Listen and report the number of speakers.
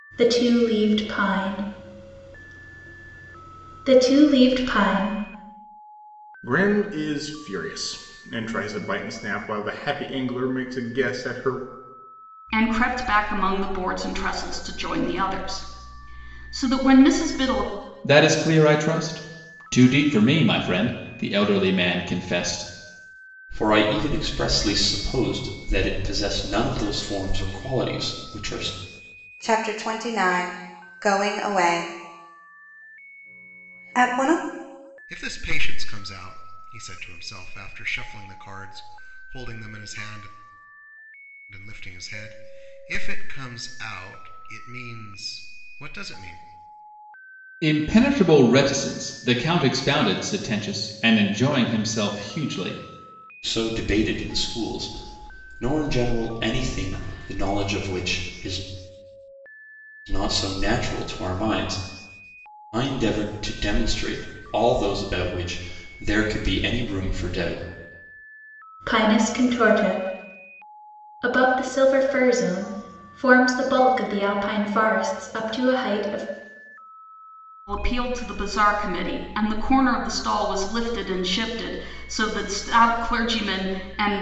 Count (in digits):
7